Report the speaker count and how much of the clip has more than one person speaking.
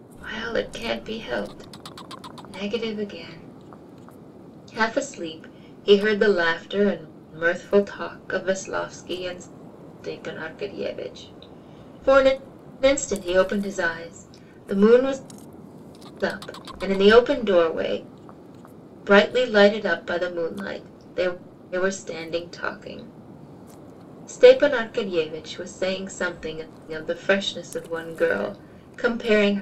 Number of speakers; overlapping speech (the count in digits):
1, no overlap